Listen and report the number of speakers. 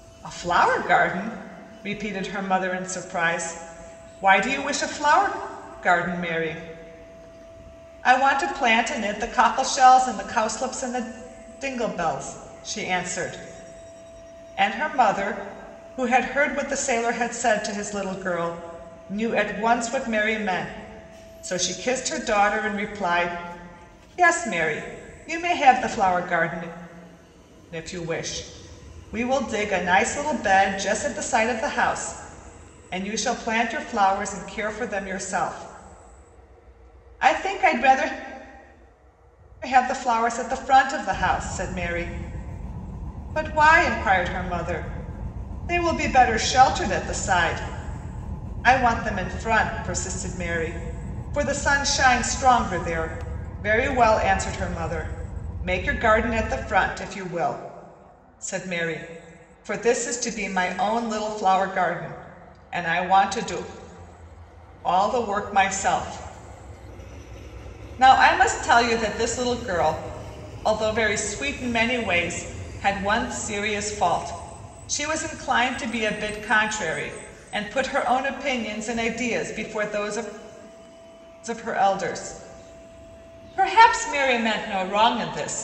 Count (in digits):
1